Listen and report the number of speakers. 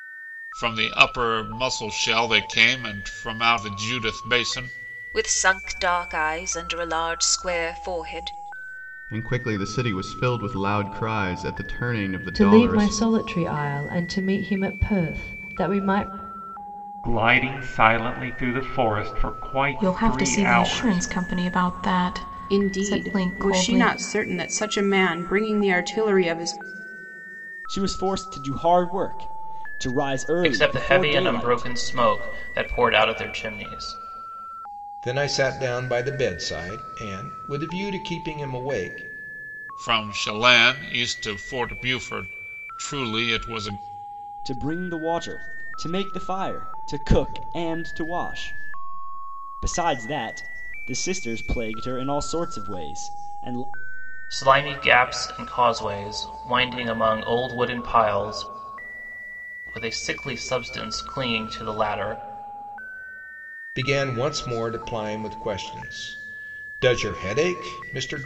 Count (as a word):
ten